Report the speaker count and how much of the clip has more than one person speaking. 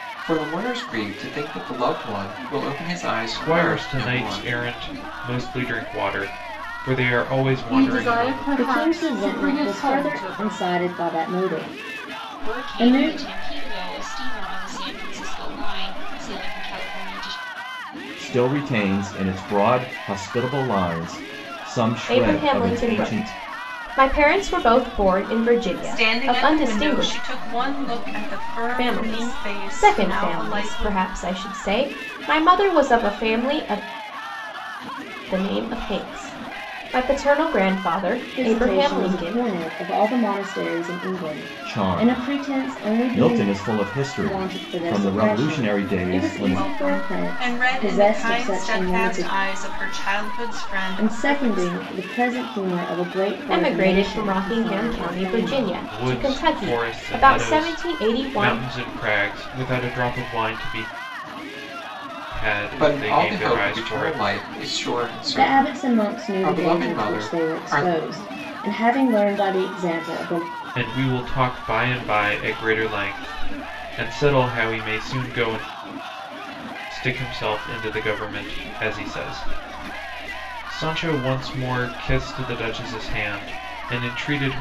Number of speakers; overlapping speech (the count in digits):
8, about 34%